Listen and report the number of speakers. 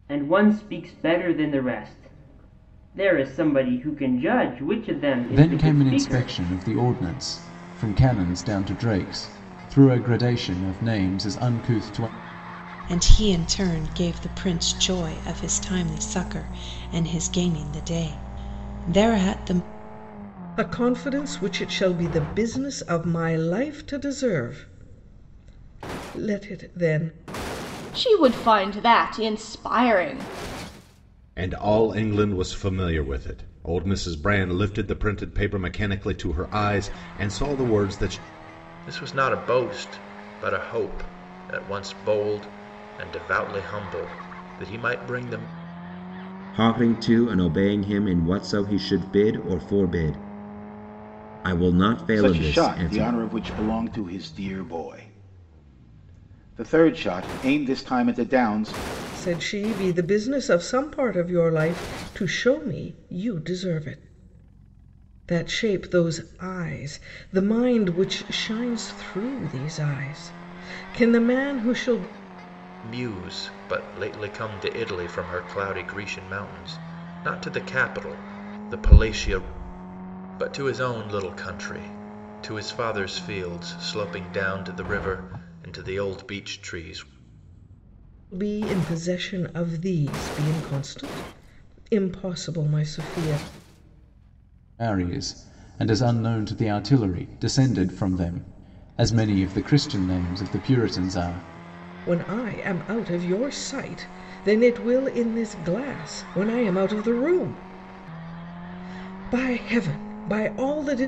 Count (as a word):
nine